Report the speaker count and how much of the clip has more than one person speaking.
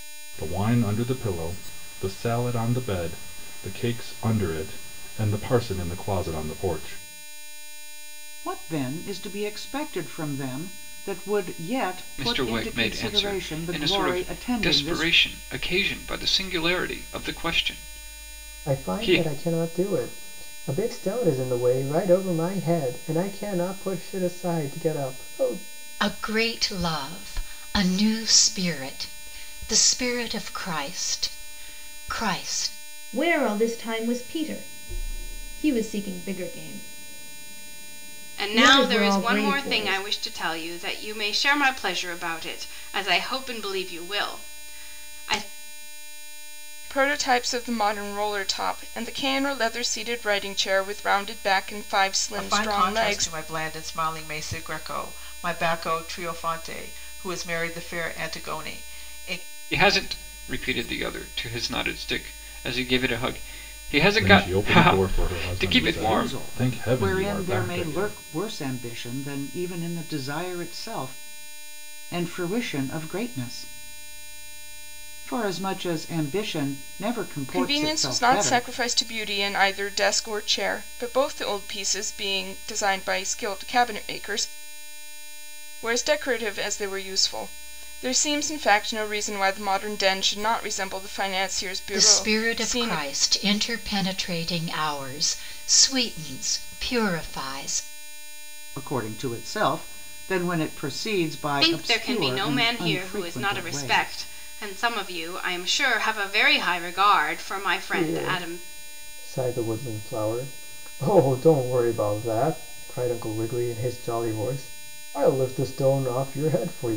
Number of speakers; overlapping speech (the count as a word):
nine, about 14%